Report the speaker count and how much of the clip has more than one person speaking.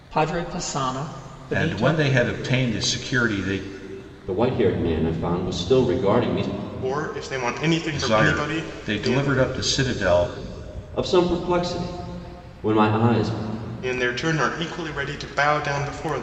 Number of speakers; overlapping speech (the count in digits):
4, about 11%